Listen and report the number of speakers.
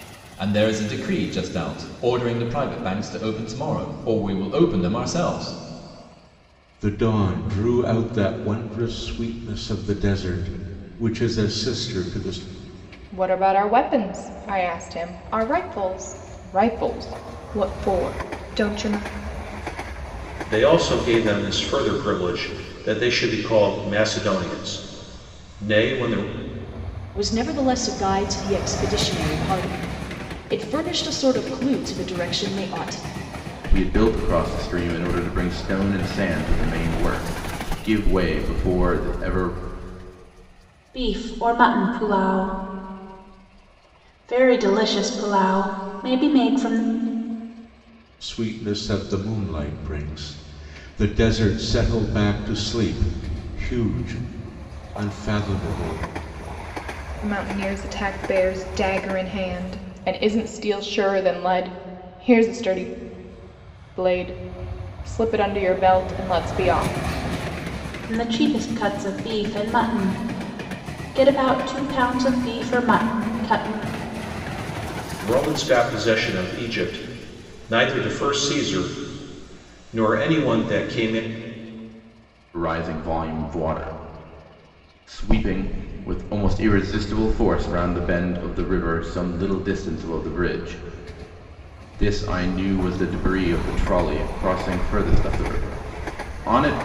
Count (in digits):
7